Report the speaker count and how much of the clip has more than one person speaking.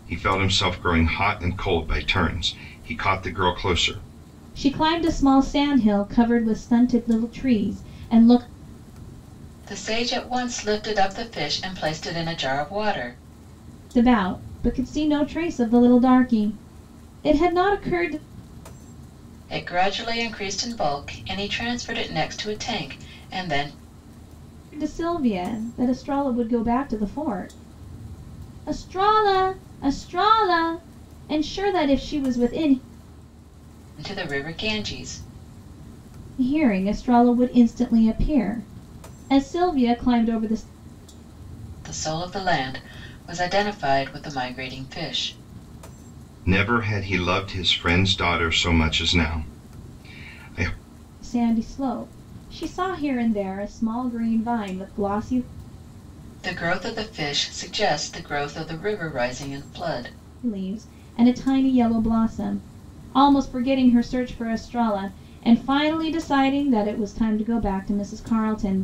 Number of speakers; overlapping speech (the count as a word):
three, no overlap